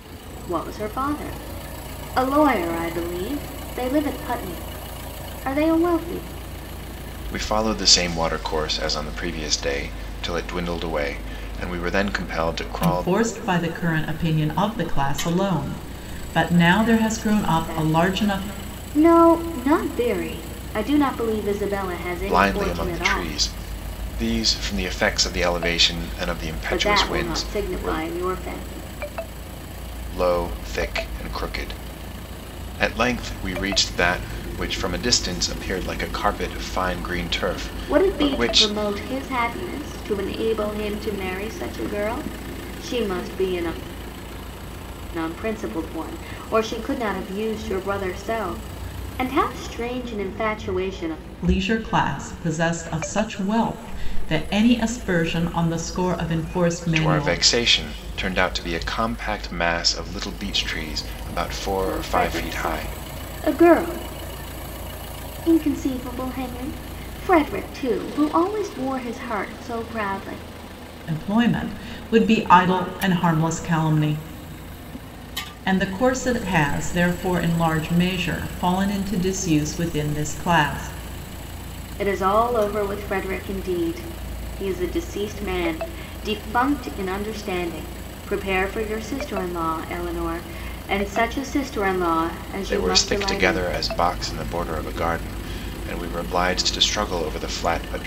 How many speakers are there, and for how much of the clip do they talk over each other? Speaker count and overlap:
3, about 8%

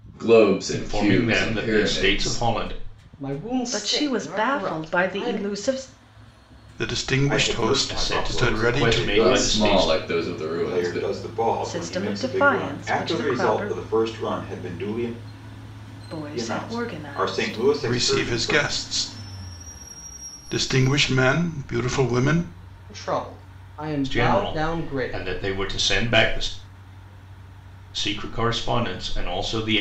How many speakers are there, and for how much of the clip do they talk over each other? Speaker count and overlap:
6, about 42%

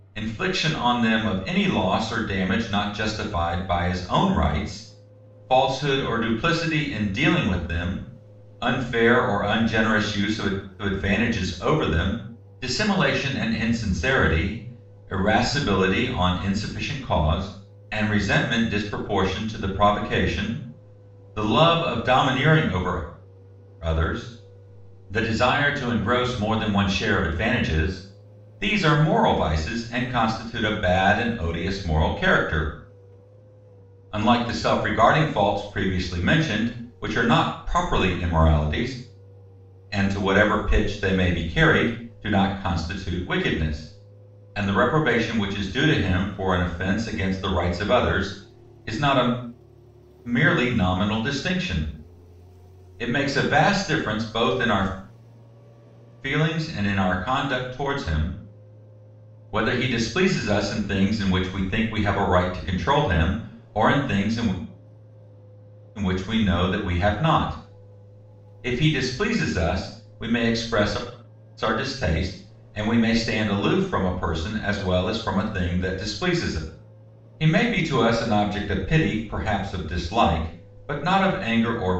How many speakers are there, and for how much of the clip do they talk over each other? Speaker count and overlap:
1, no overlap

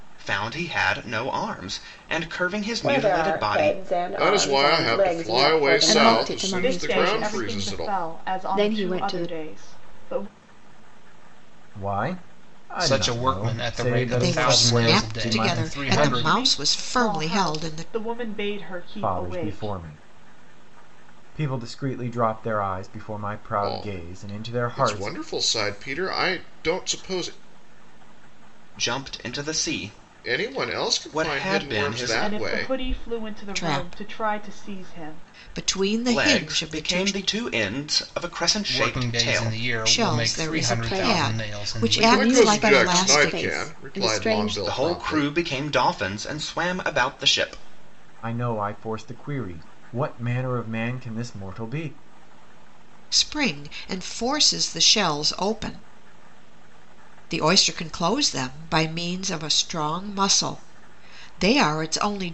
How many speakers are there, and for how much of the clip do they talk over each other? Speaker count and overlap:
8, about 41%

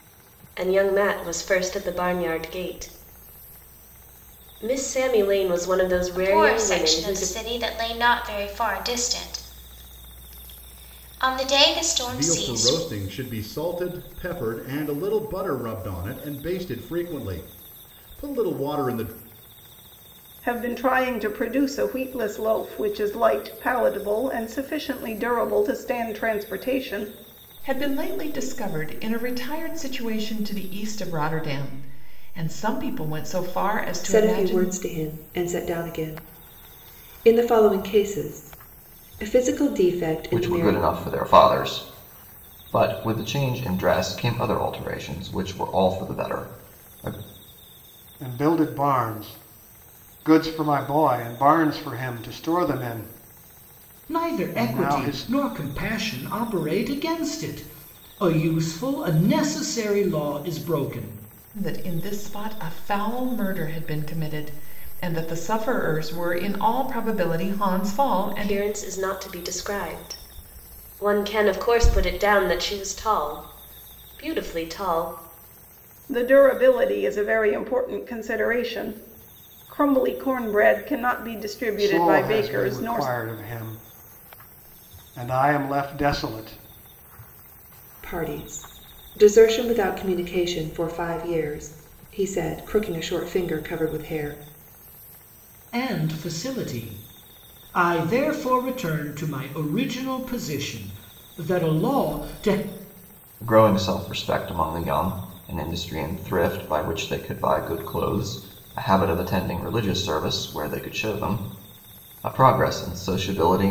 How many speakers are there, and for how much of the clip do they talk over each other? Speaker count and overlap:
9, about 5%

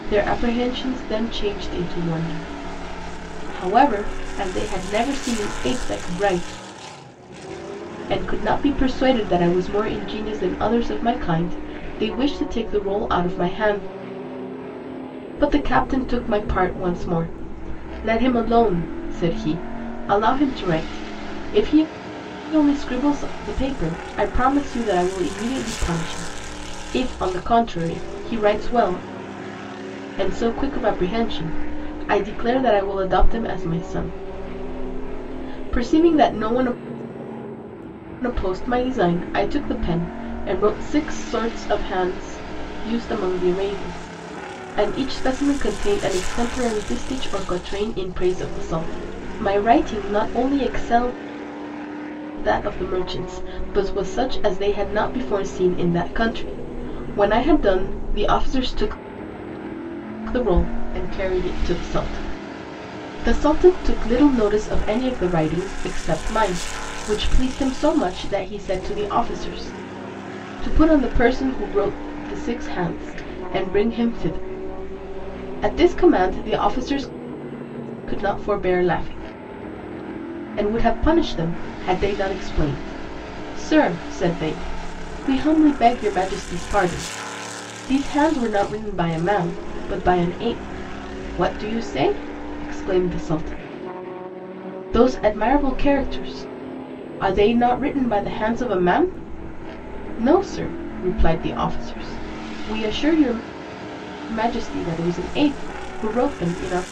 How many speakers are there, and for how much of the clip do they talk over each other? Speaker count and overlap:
1, no overlap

